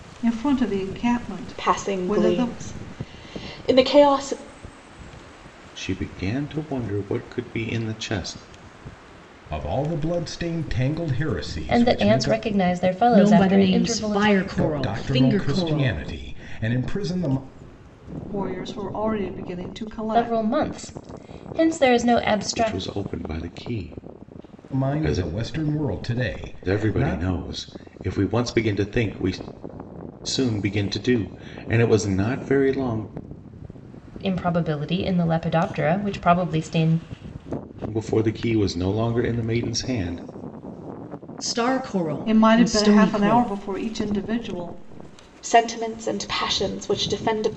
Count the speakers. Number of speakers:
six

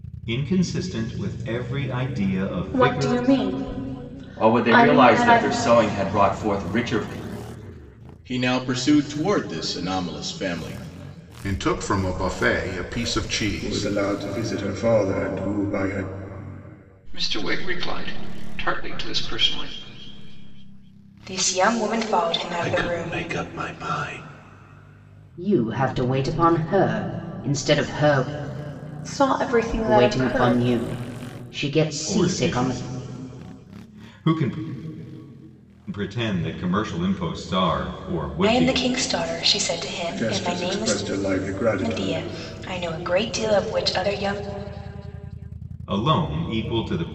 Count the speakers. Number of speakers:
ten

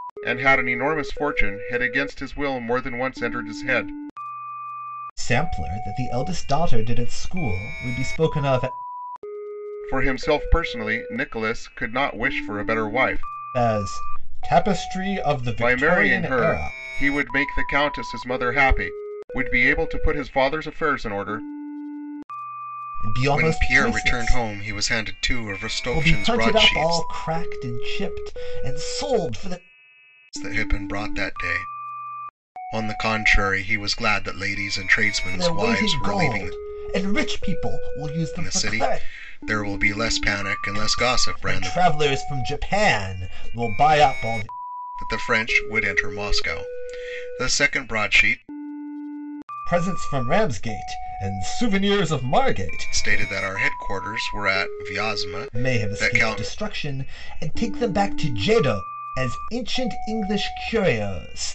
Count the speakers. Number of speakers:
two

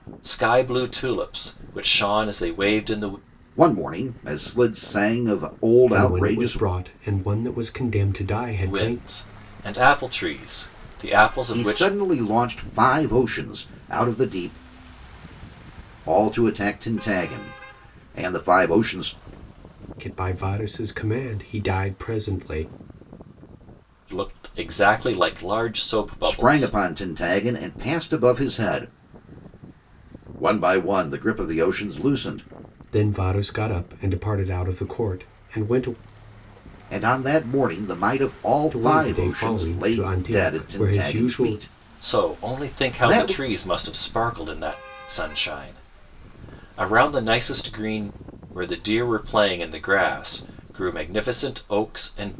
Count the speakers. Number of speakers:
three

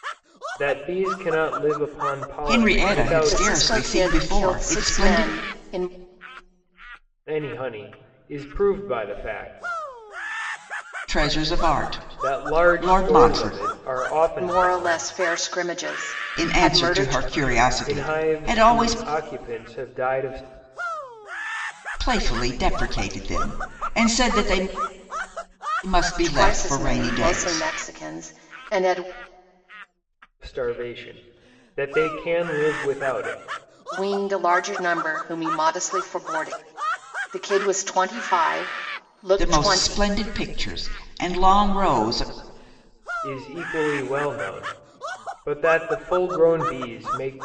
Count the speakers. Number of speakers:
three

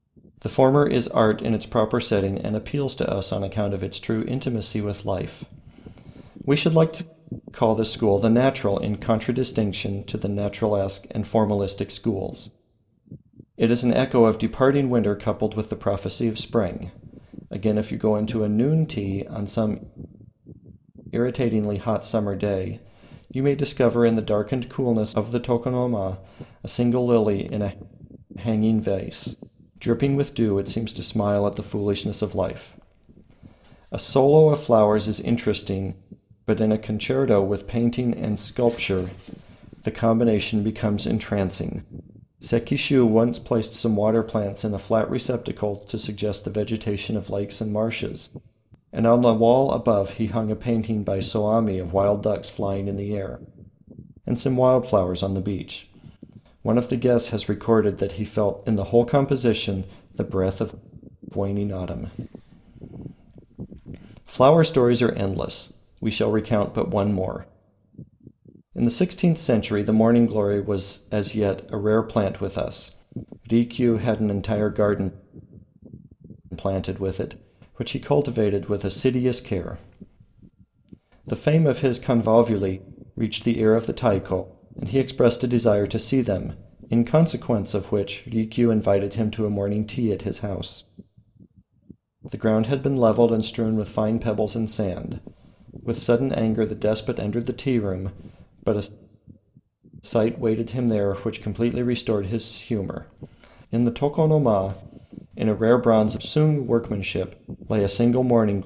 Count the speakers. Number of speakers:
one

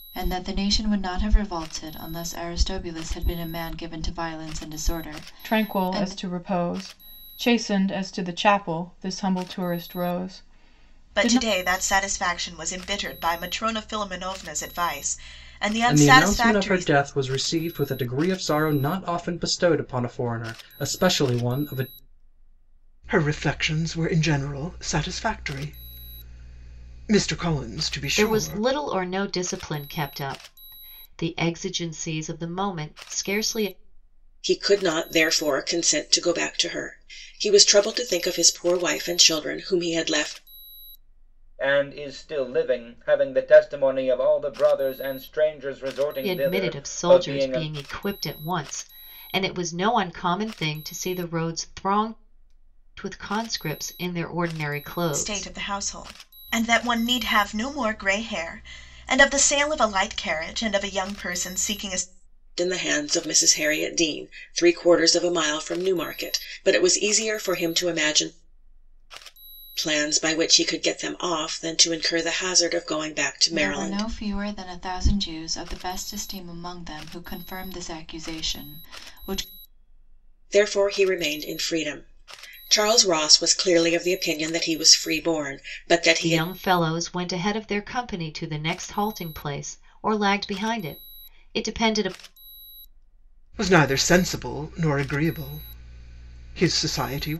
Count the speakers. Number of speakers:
eight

